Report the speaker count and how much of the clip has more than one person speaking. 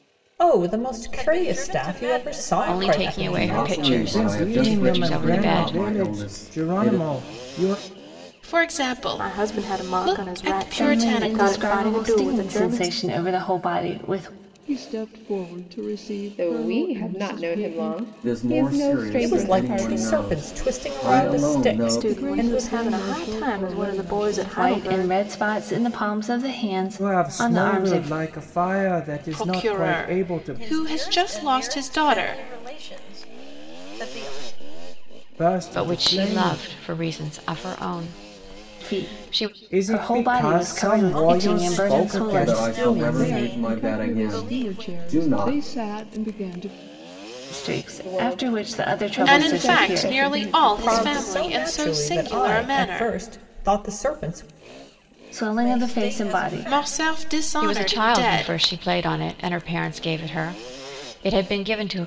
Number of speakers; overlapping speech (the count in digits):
10, about 61%